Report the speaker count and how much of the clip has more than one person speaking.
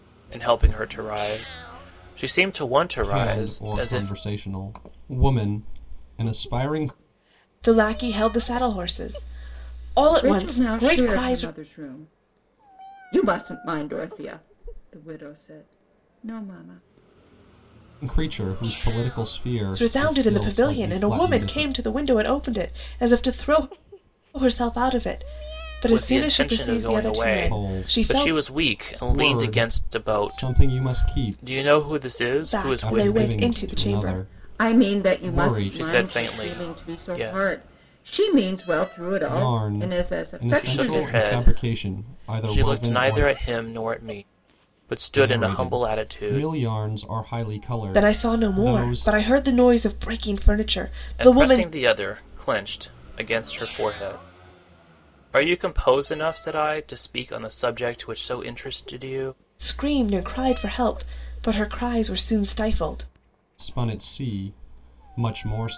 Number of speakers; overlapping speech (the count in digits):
4, about 34%